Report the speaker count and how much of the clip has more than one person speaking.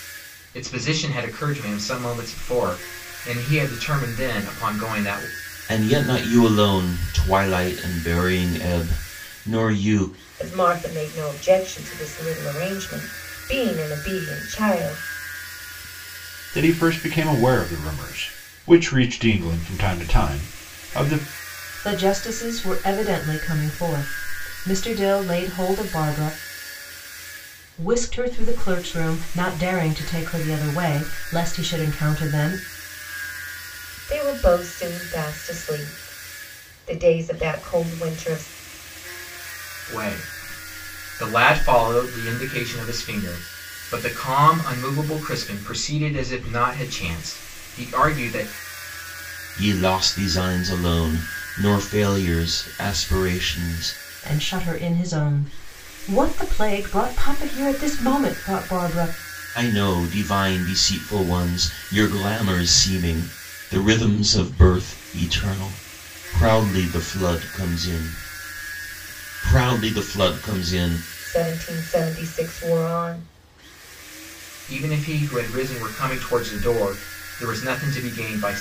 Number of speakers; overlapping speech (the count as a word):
five, no overlap